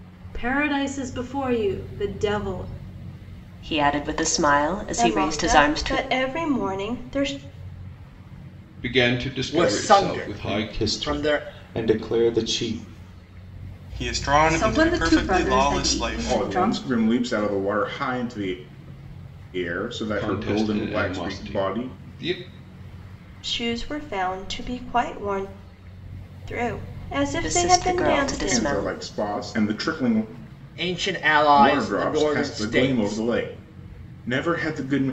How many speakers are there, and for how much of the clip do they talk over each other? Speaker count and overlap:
9, about 30%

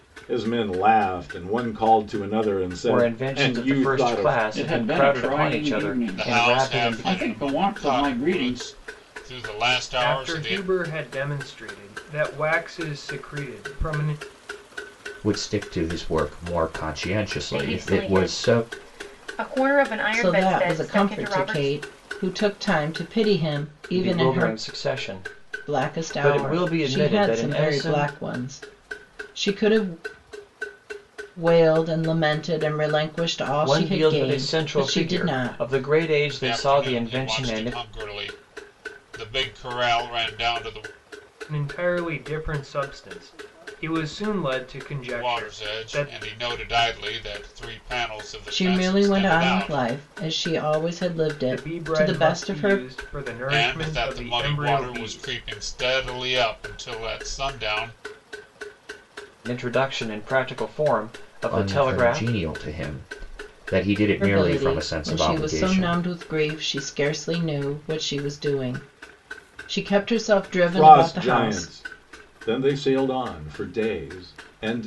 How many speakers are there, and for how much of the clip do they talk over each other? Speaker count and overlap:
8, about 33%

